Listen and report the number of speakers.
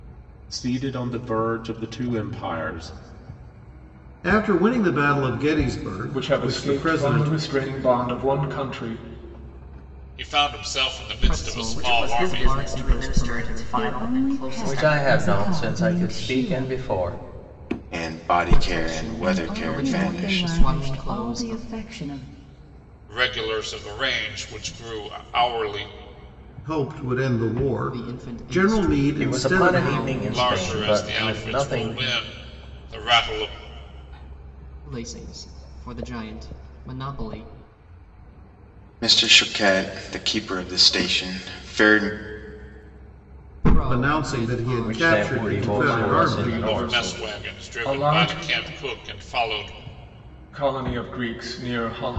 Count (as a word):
nine